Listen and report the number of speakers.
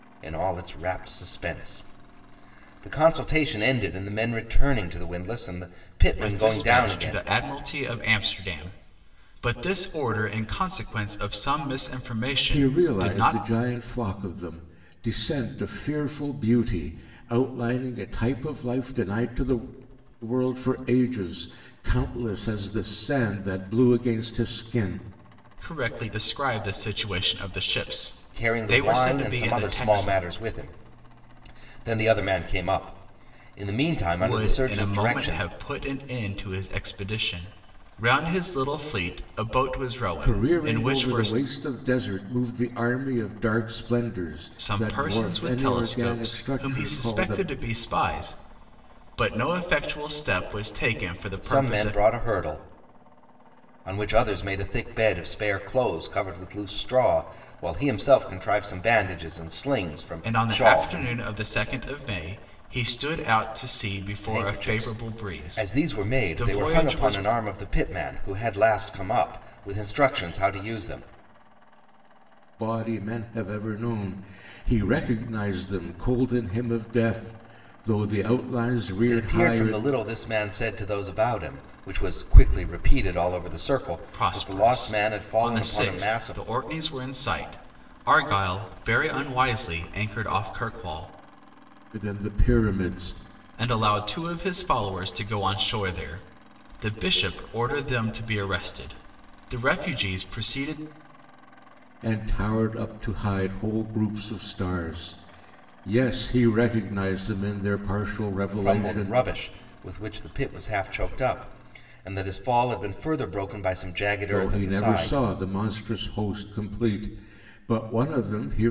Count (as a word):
three